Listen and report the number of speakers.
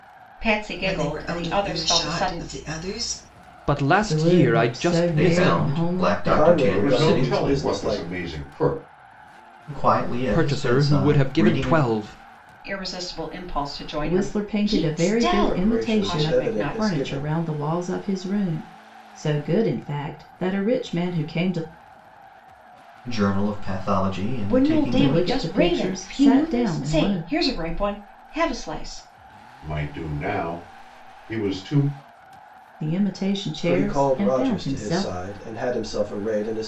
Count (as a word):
seven